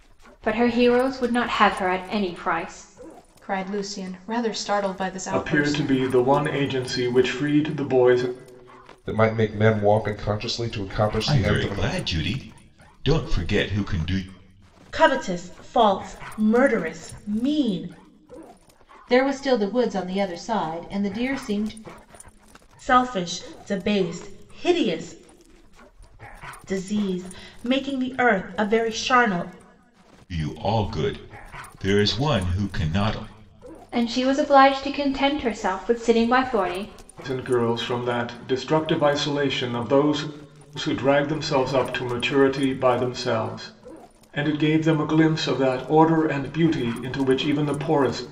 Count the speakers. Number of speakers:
7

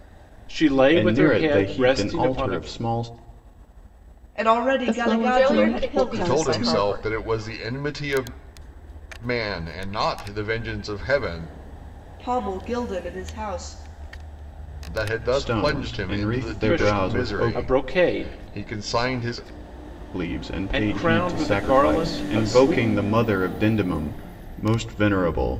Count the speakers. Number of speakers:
6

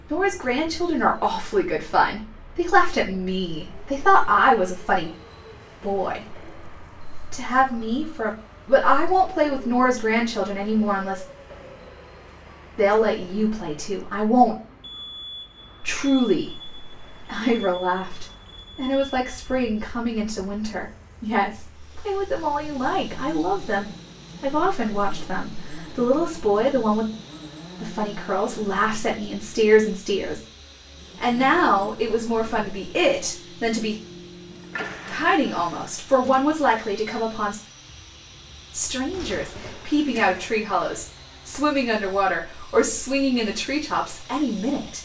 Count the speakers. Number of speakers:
1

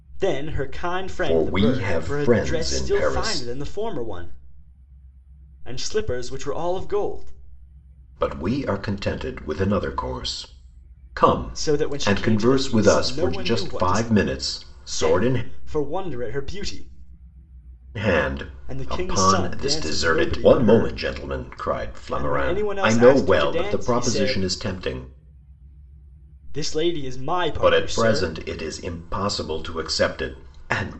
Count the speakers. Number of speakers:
2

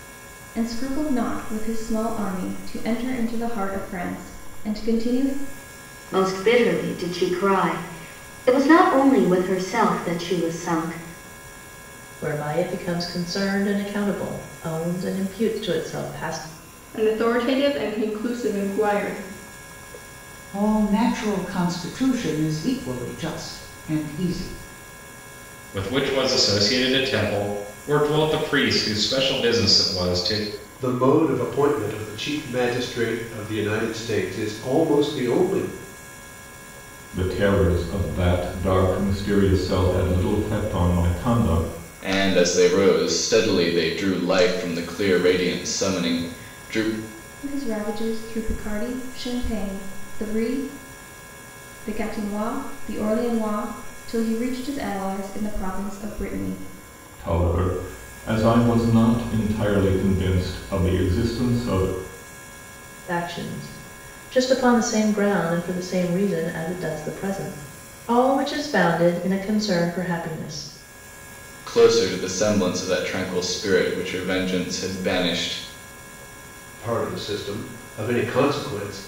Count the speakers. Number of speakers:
9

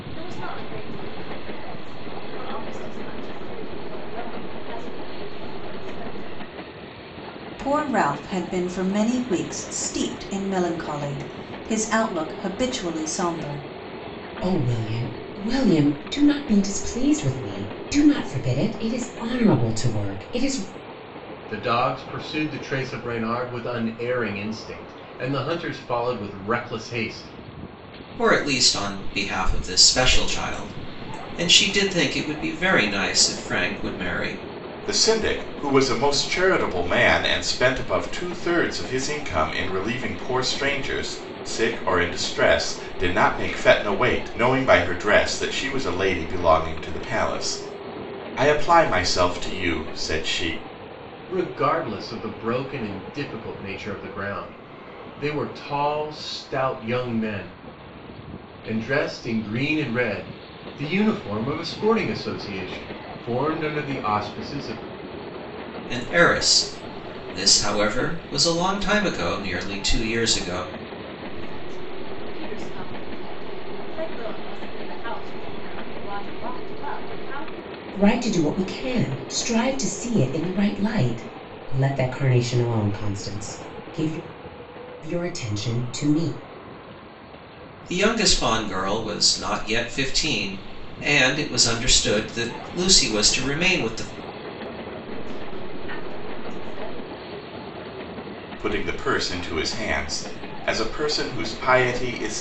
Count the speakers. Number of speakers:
6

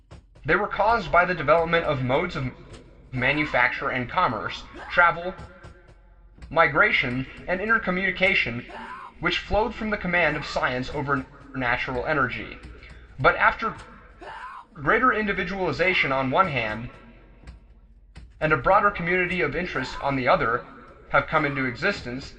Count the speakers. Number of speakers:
1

